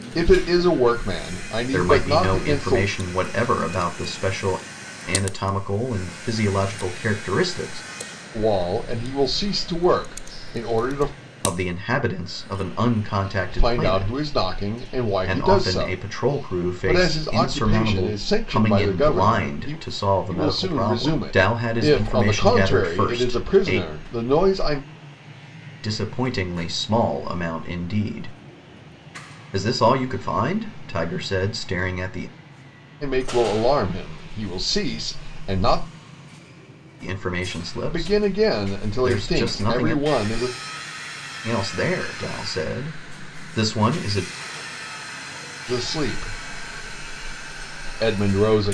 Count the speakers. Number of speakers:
2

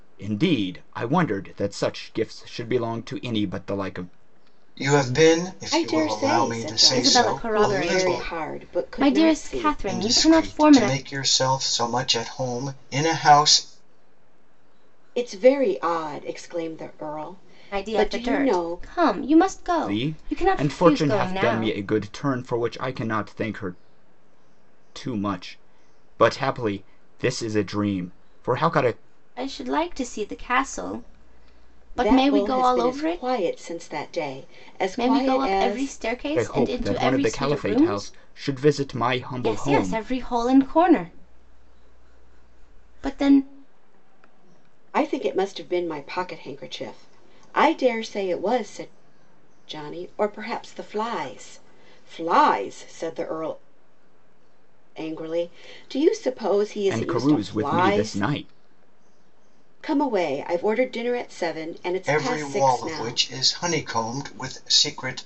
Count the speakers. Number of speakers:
4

